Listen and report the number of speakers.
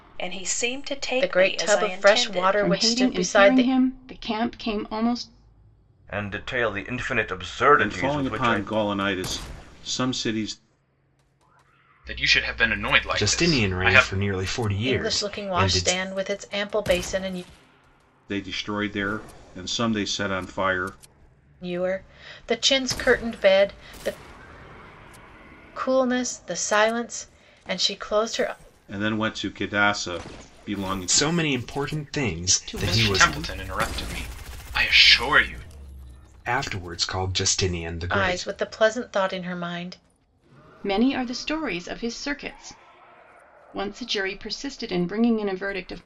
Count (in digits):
7